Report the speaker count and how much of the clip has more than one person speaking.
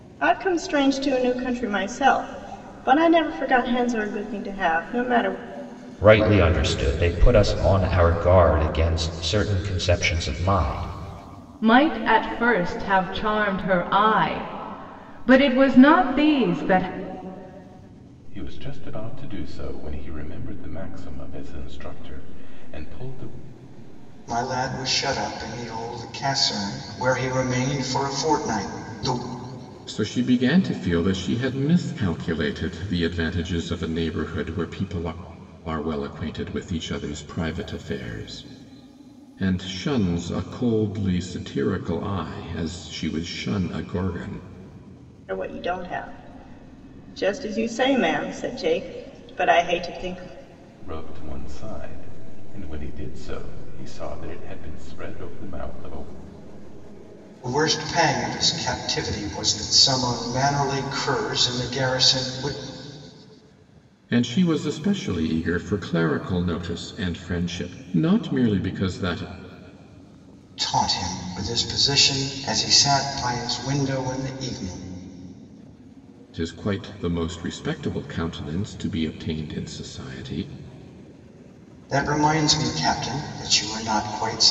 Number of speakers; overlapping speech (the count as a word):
six, no overlap